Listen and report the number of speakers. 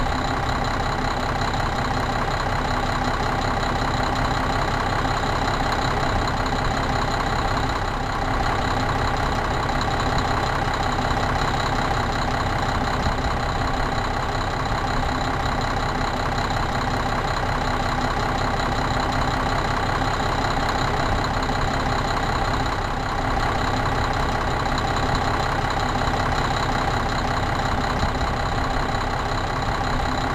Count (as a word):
zero